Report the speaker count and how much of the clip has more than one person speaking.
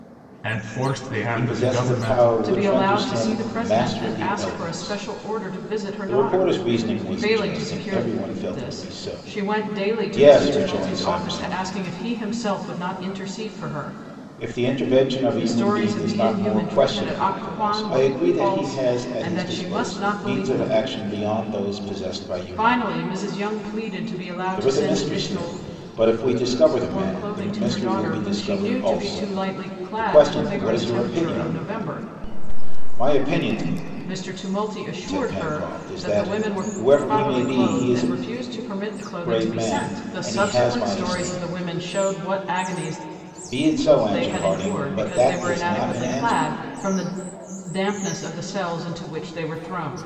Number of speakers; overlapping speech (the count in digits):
2, about 58%